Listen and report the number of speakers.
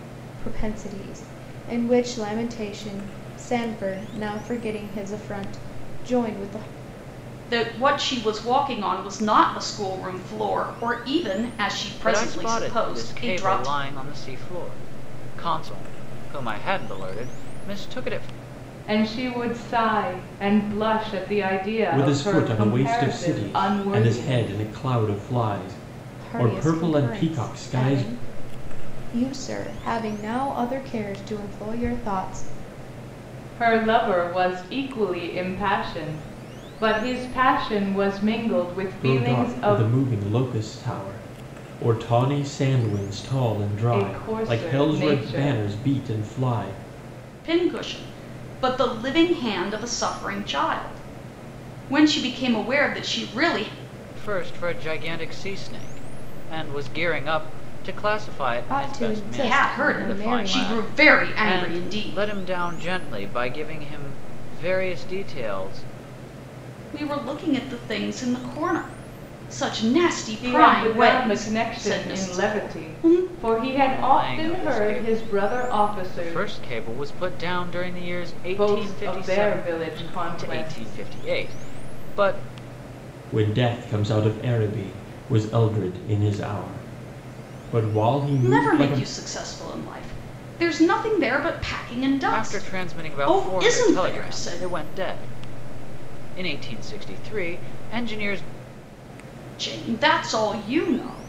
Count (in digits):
5